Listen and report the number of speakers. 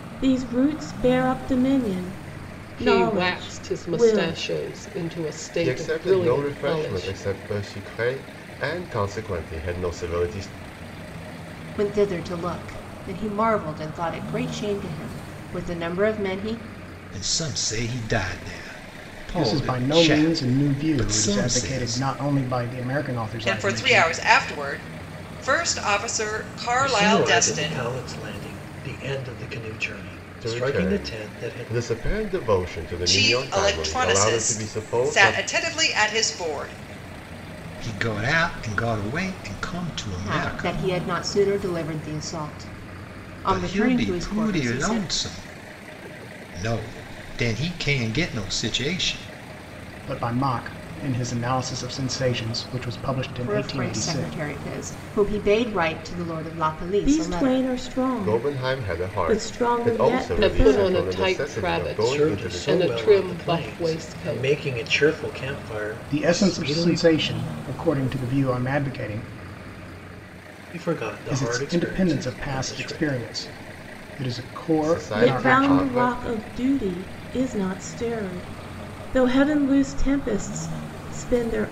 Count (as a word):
eight